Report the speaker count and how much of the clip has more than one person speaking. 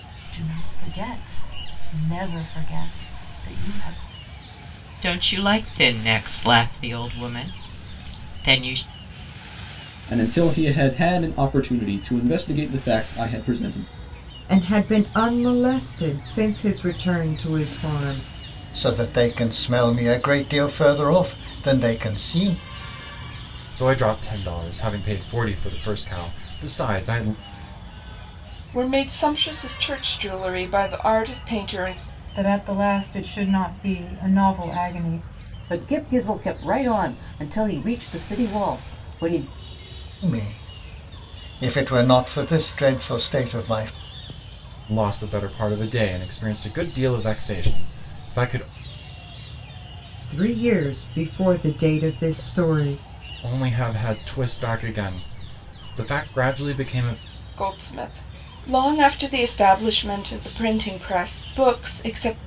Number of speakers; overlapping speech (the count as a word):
nine, no overlap